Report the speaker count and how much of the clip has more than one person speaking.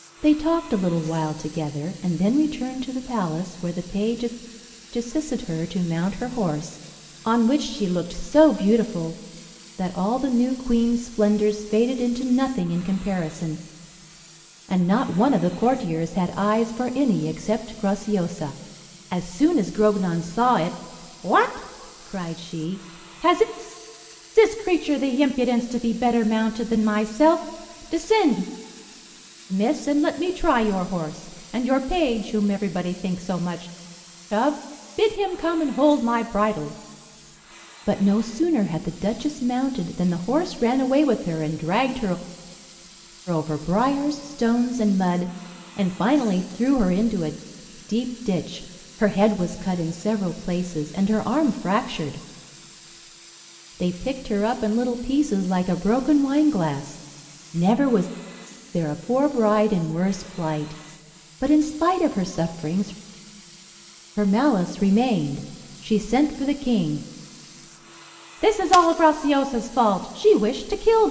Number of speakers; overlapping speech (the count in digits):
1, no overlap